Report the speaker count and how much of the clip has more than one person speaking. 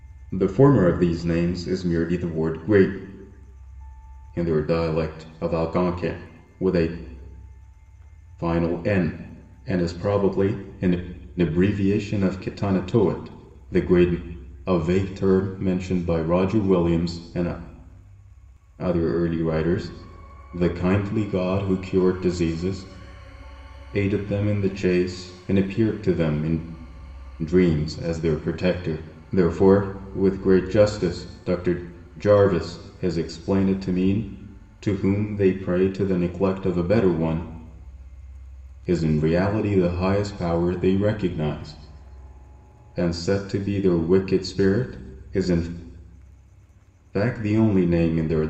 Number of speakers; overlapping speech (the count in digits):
1, no overlap